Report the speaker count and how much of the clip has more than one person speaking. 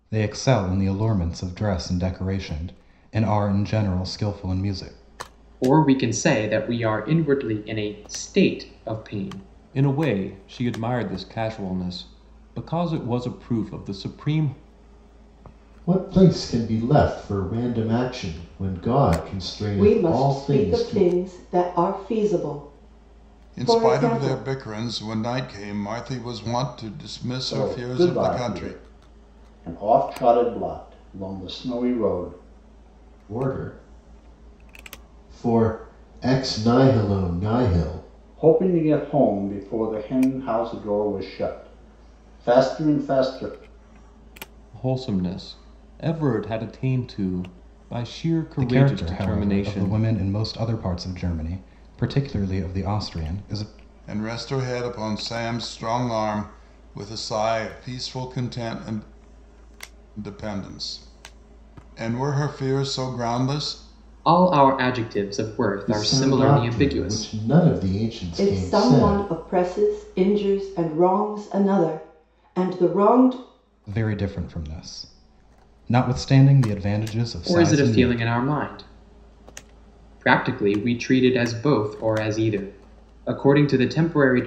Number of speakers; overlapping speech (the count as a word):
seven, about 10%